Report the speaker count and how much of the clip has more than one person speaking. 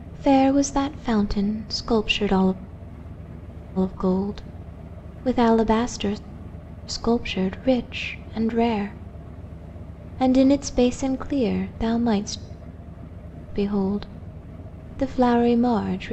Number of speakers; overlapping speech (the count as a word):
one, no overlap